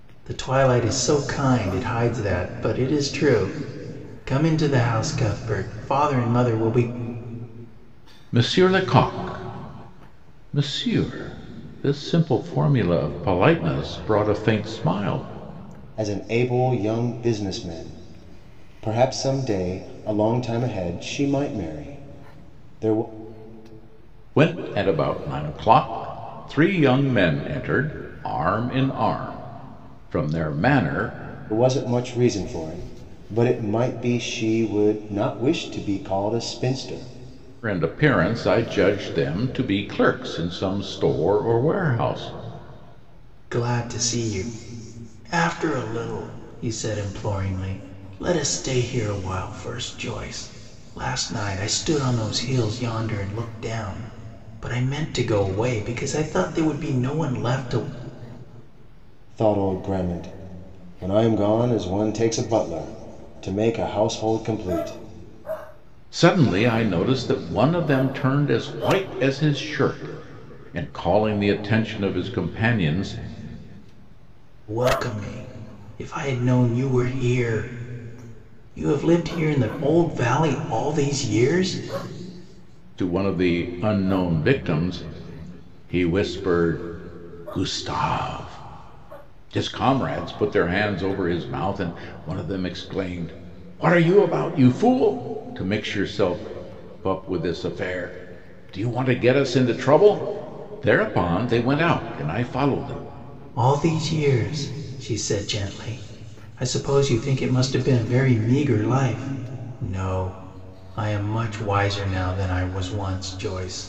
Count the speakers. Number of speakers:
3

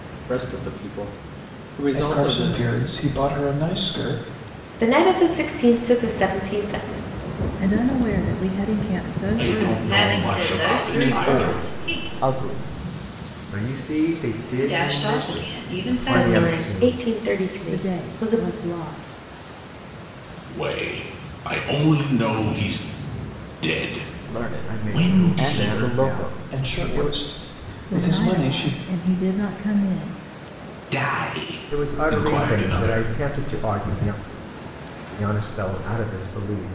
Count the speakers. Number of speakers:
8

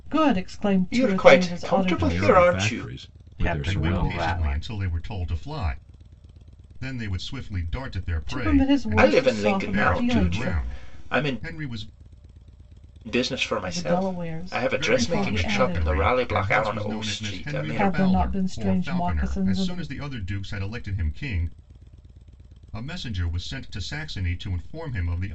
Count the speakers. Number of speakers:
5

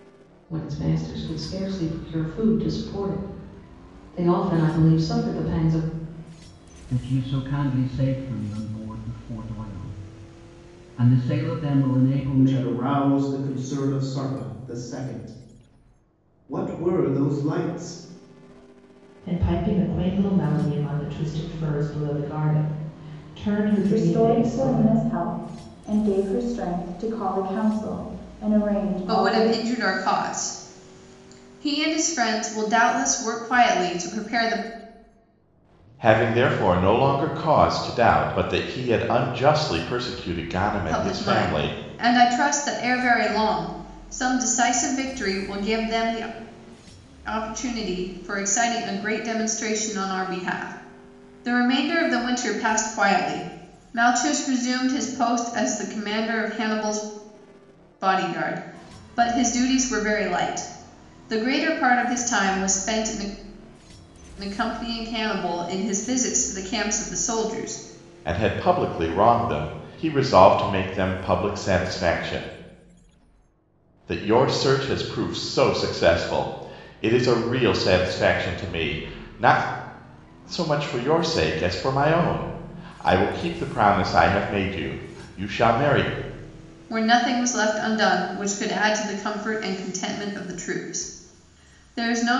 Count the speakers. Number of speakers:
7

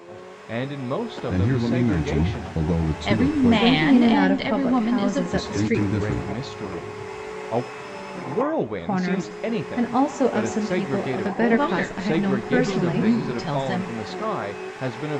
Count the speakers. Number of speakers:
4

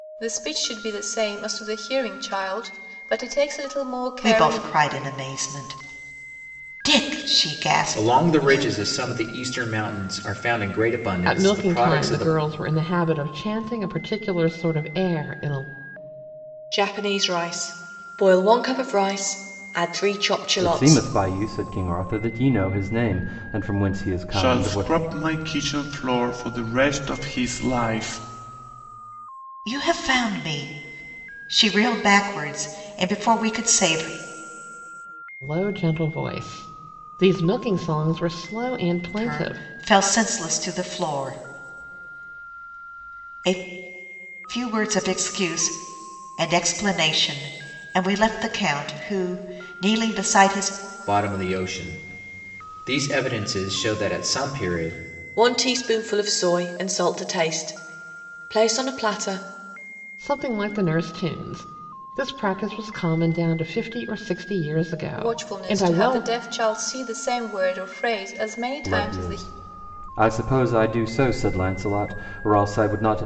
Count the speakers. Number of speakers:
7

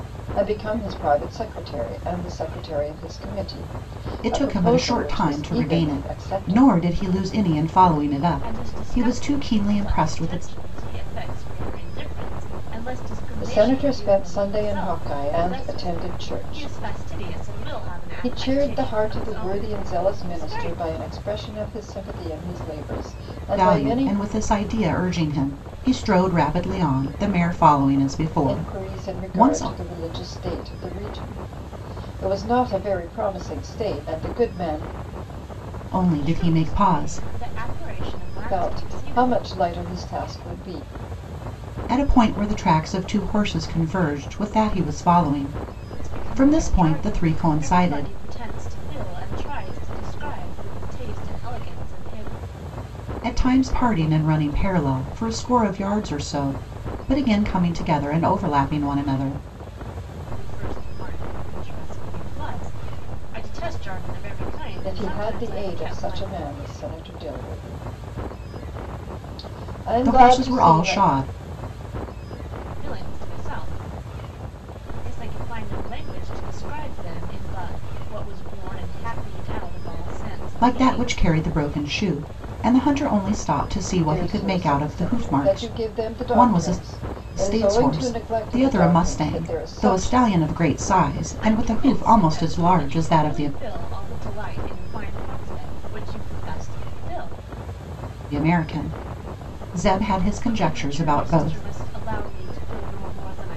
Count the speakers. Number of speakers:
3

